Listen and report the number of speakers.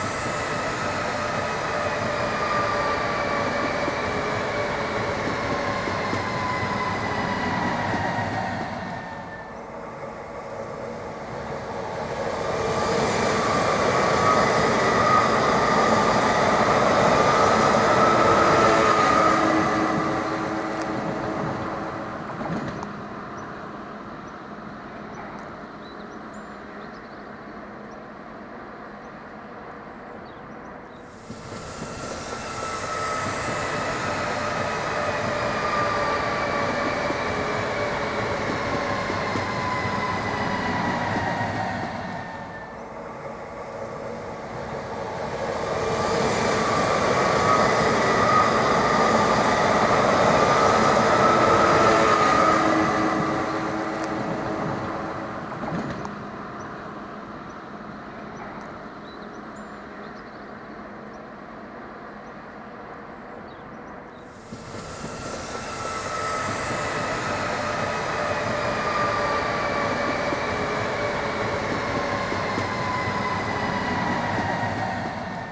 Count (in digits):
0